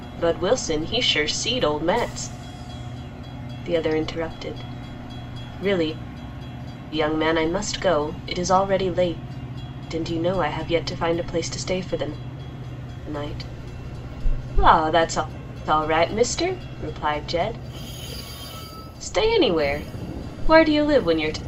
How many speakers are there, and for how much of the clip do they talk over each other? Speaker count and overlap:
1, no overlap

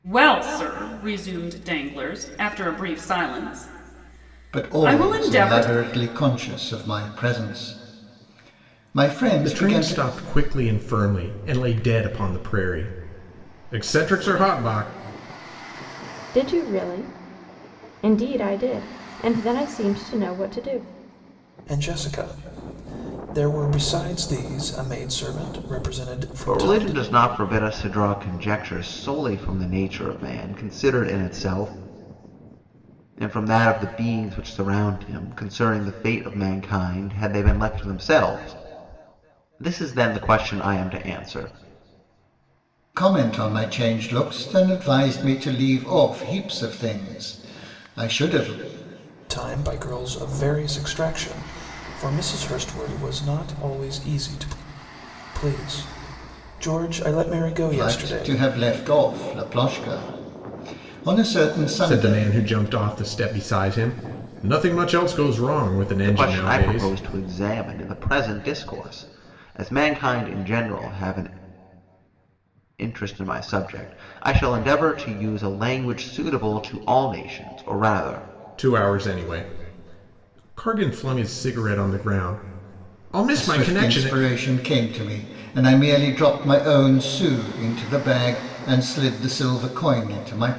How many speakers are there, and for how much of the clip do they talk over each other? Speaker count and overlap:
6, about 6%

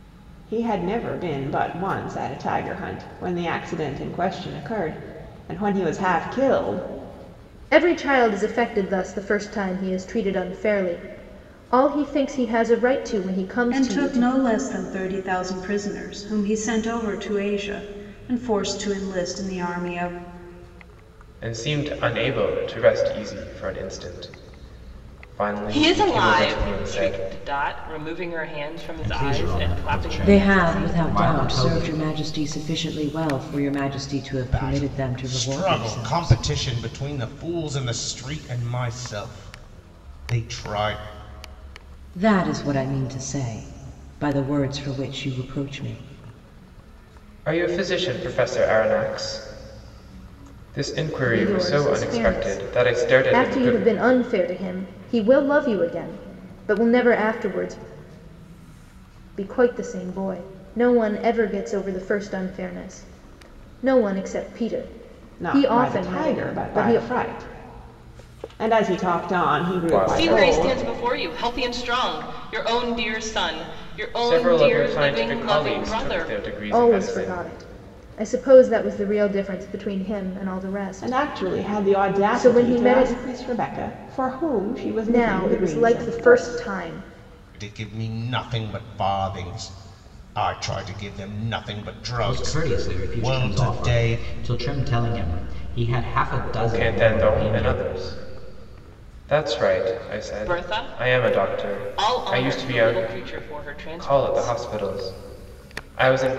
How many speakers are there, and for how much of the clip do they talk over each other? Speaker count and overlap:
8, about 24%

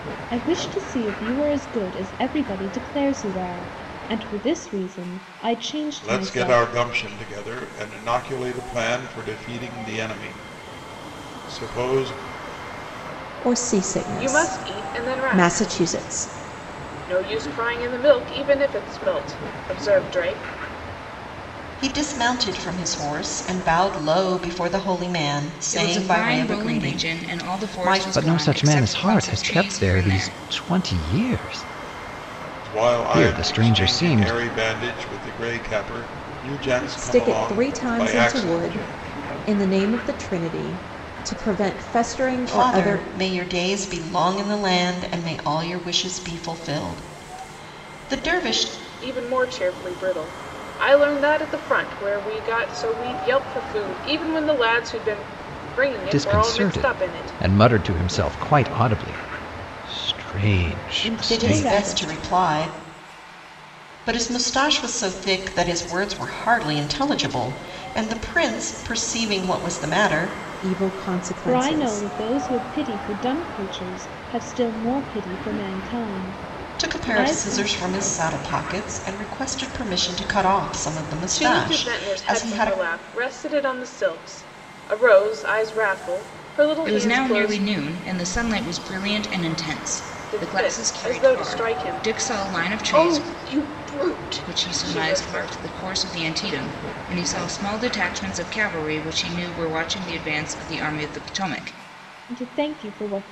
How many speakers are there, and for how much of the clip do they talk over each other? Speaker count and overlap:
7, about 22%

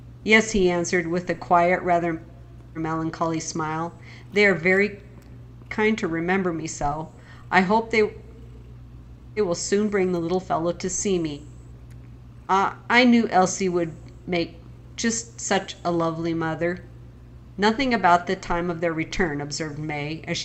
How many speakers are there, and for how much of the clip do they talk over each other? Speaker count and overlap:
1, no overlap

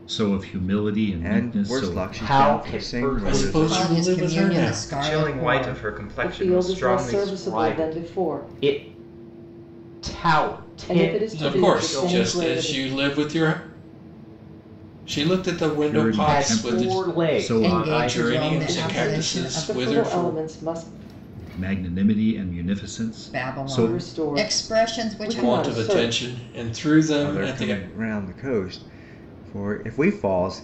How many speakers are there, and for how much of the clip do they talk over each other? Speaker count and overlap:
7, about 55%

